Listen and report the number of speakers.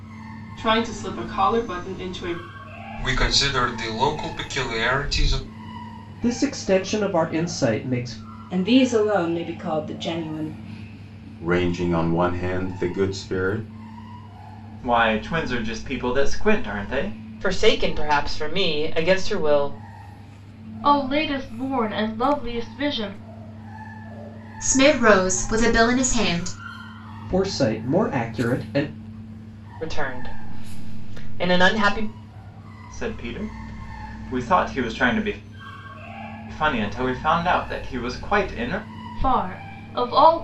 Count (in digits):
9